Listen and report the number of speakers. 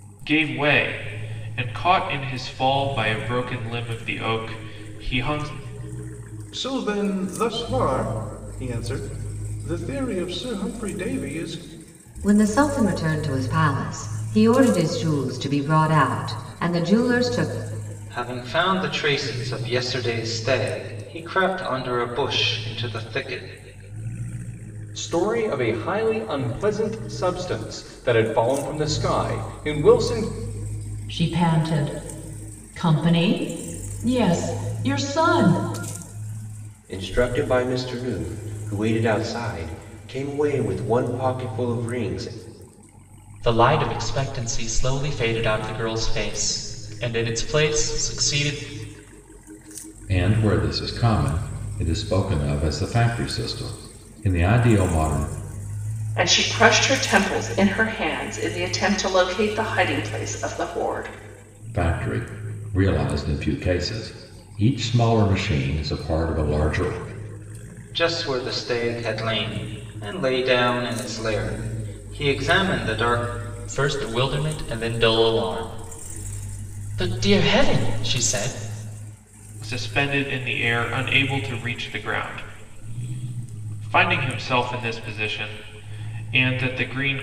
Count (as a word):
ten